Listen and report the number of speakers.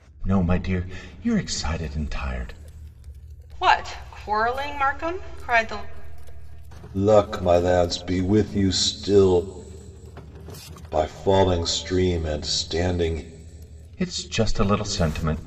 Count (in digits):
3